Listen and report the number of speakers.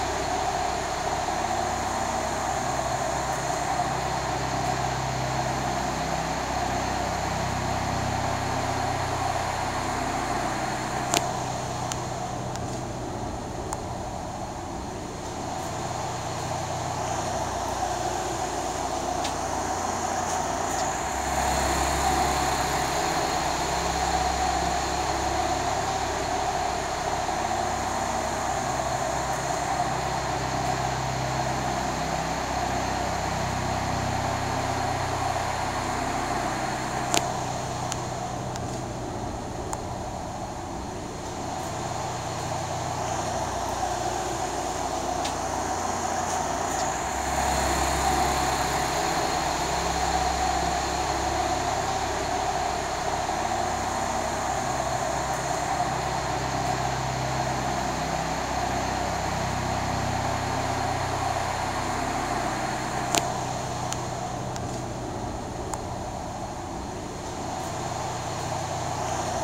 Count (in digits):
0